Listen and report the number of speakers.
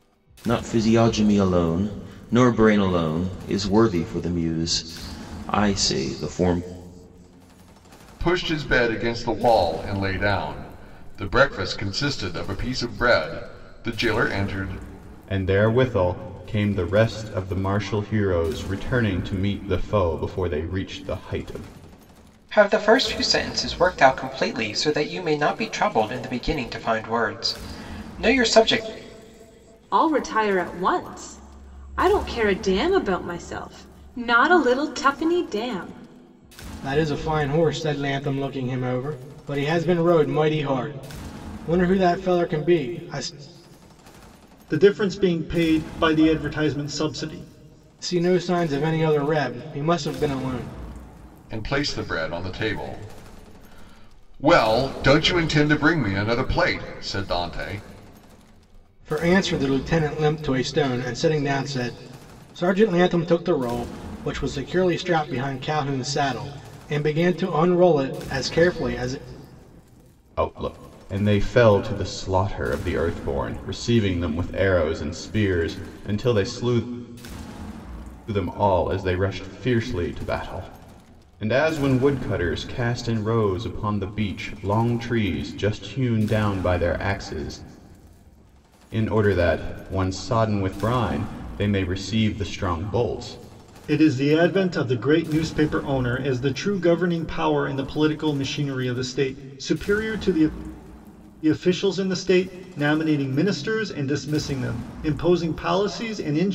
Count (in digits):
7